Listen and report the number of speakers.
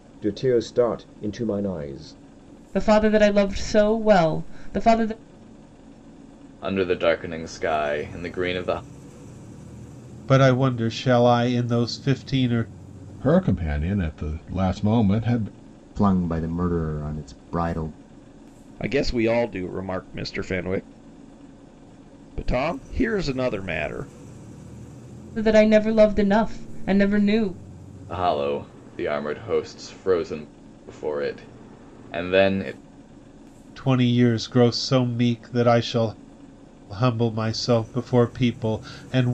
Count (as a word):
seven